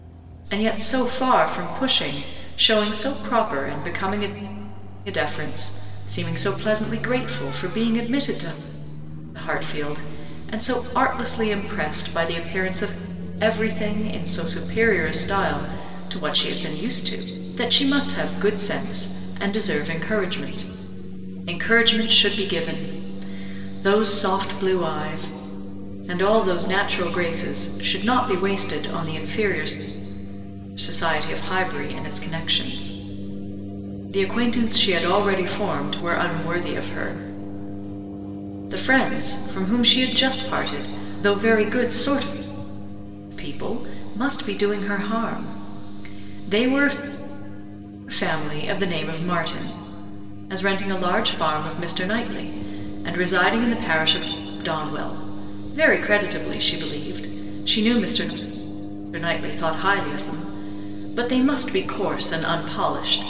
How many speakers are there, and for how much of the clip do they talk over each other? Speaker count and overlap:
one, no overlap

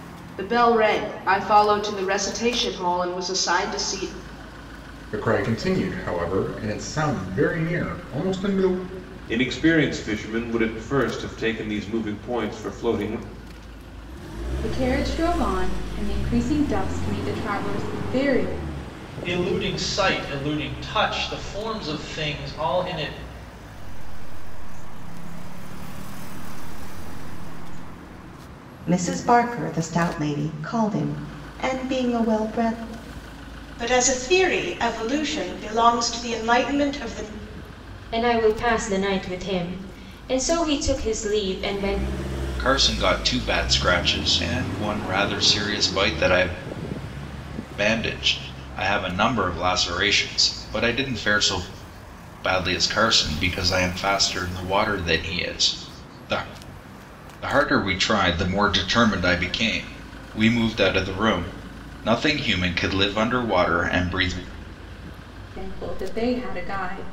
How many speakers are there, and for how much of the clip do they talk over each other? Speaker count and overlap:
ten, no overlap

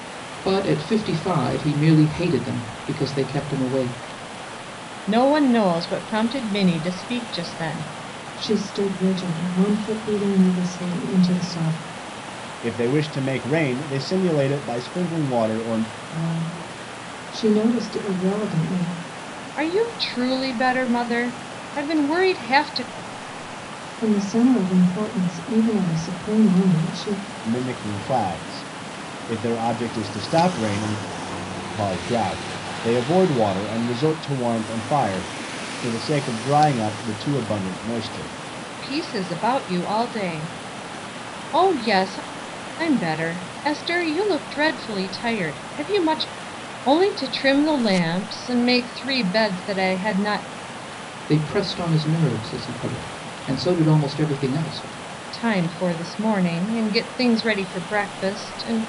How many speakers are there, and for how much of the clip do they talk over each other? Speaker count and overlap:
four, no overlap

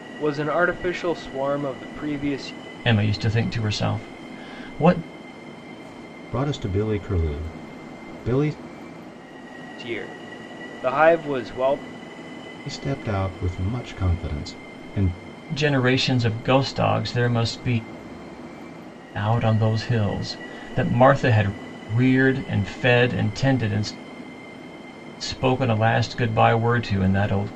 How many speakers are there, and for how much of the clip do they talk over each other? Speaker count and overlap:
three, no overlap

